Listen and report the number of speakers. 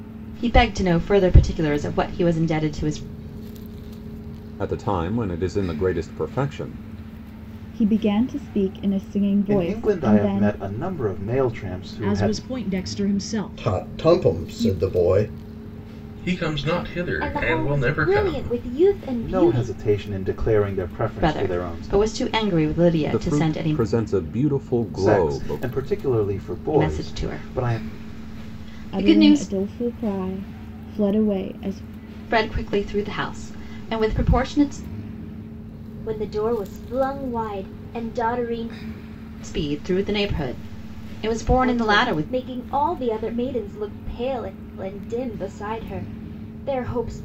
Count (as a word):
eight